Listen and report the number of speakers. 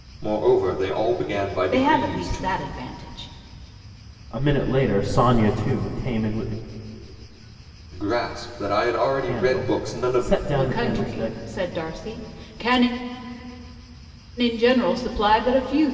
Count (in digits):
3